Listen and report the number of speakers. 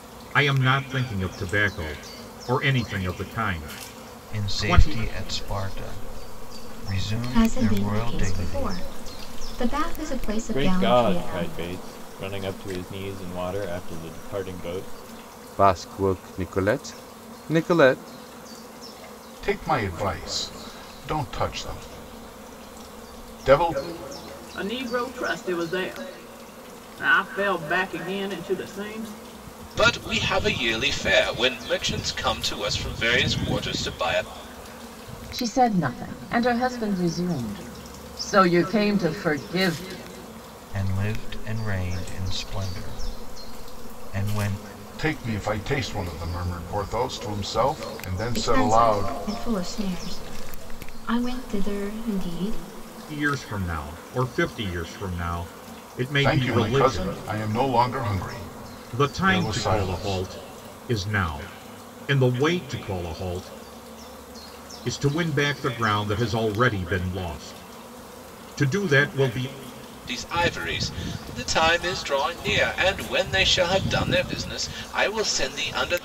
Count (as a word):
nine